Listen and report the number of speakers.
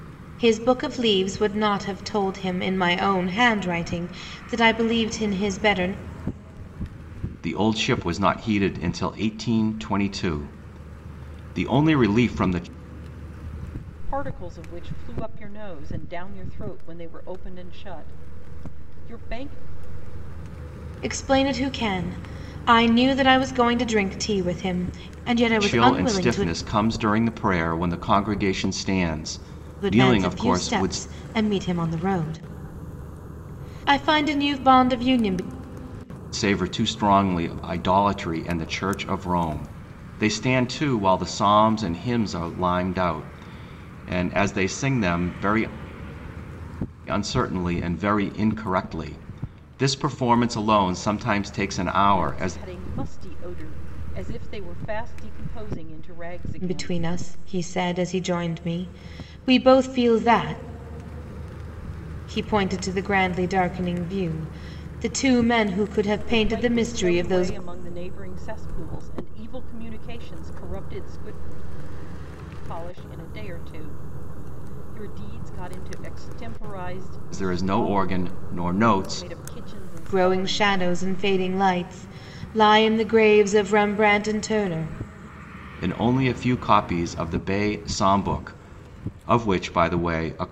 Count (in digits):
3